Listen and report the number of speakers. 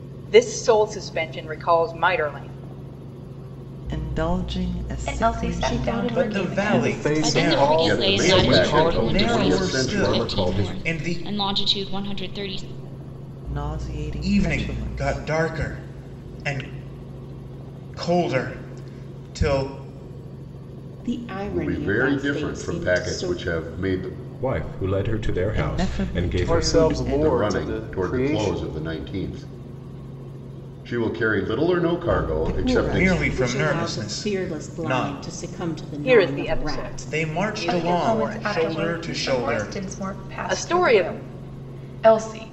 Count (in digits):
9